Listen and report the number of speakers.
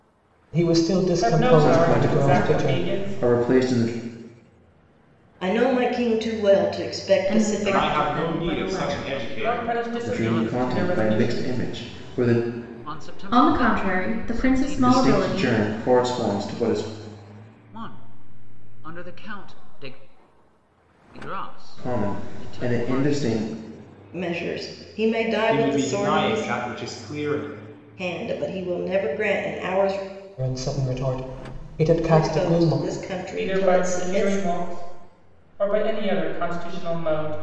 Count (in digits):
7